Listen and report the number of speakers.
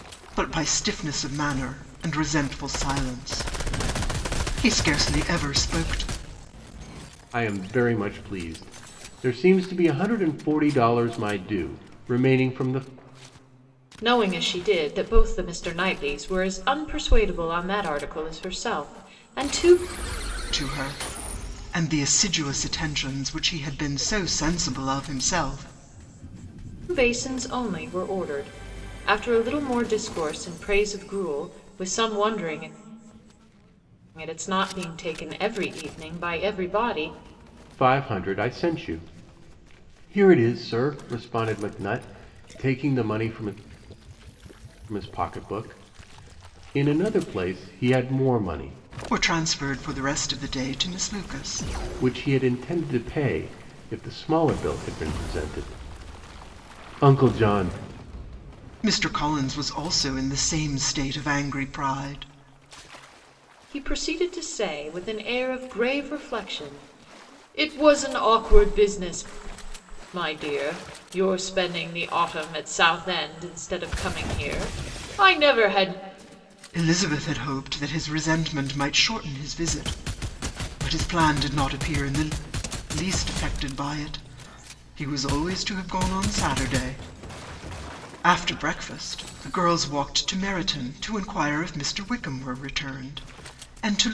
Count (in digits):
3